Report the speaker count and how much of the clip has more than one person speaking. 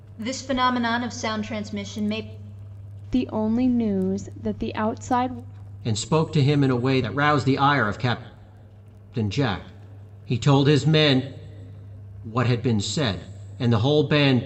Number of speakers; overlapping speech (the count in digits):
3, no overlap